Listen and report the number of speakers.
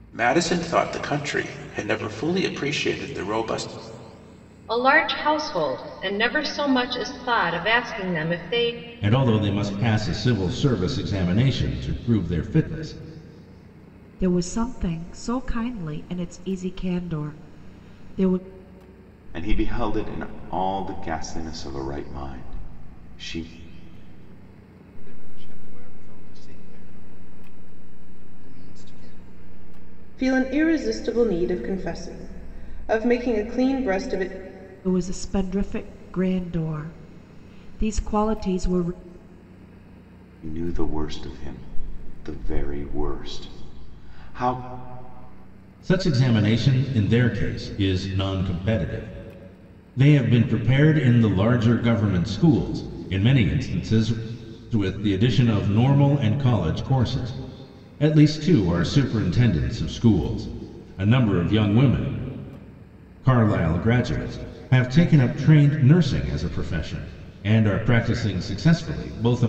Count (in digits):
7